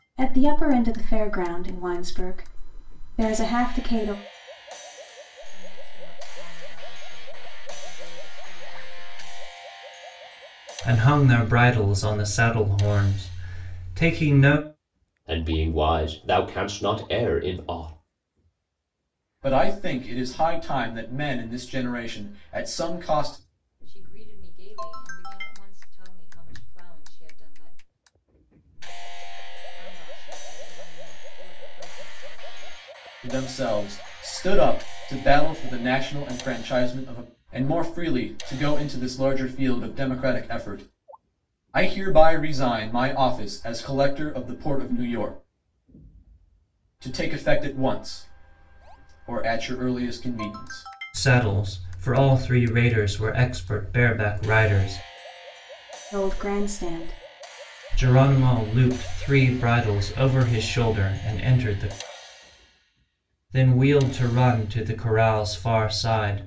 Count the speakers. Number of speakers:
five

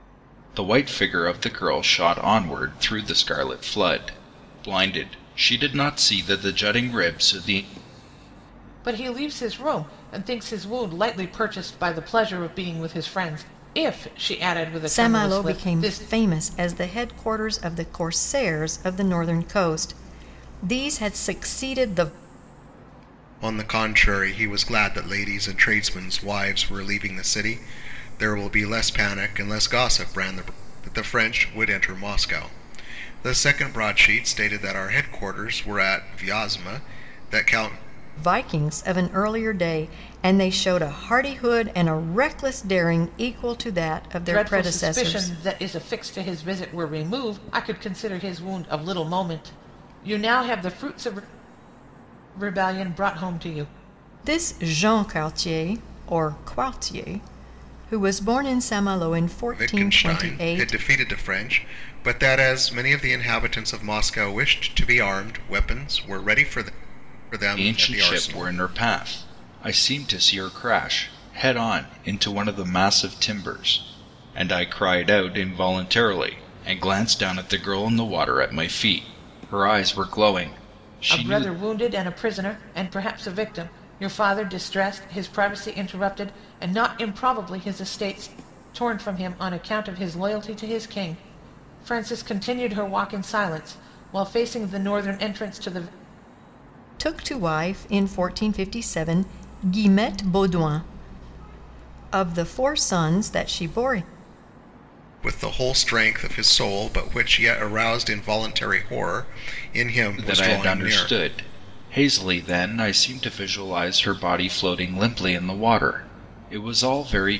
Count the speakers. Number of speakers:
four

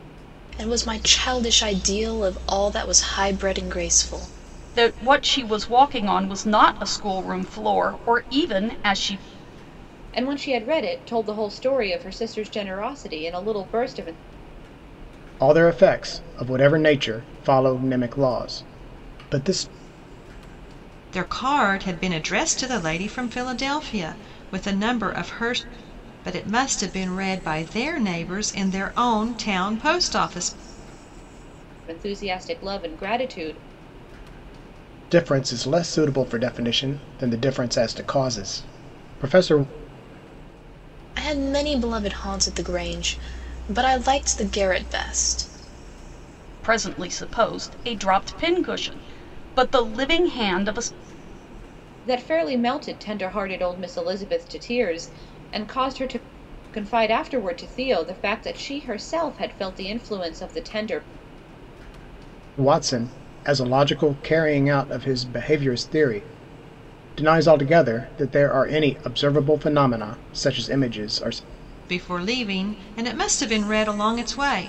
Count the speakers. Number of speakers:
five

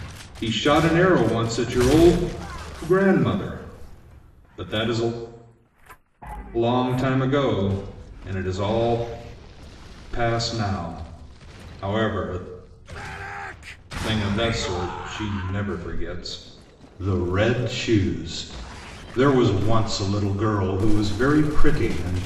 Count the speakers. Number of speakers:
one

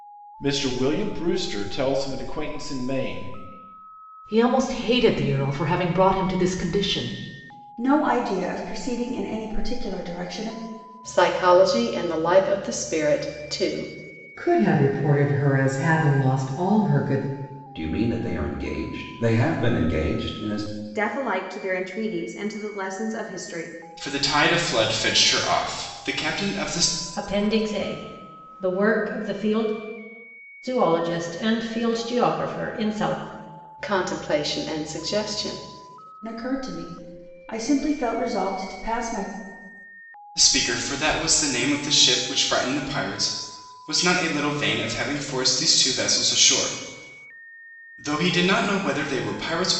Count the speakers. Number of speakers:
nine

